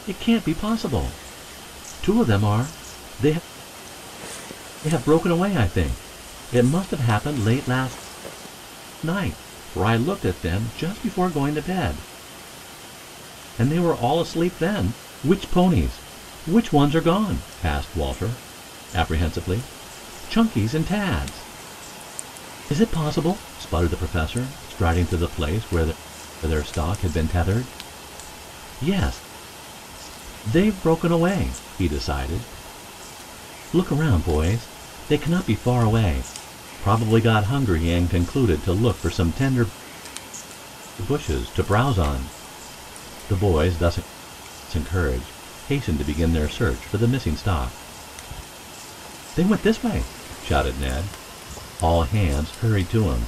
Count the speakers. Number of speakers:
1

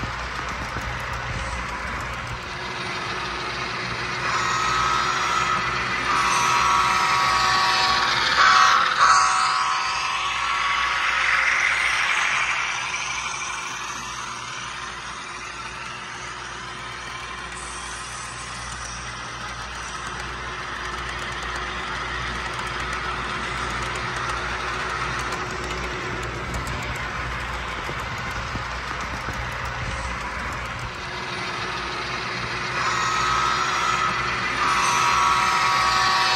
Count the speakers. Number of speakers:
0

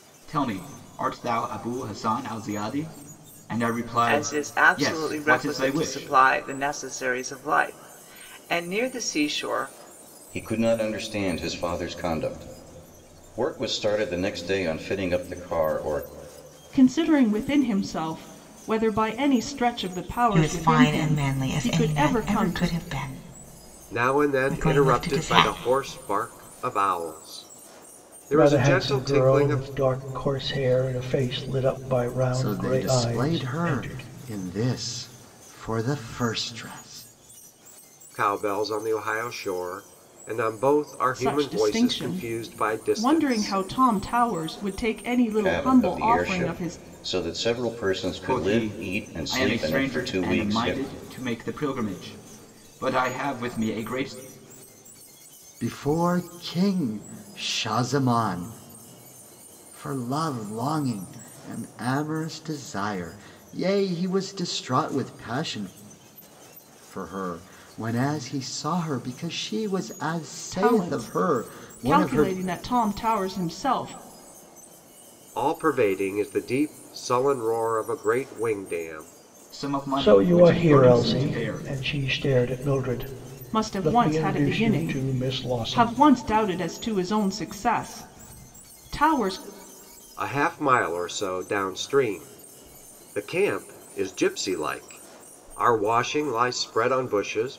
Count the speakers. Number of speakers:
8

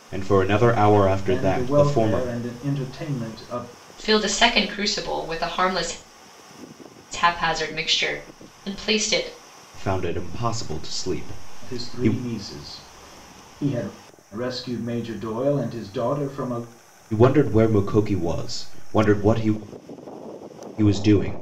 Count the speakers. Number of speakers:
3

